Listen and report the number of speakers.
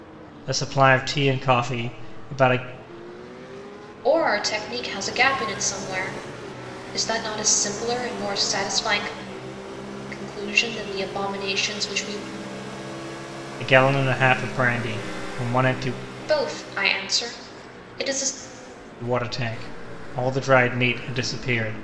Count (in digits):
2